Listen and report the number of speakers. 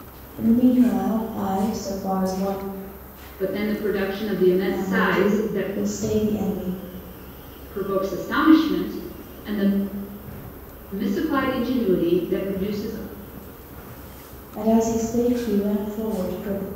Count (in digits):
2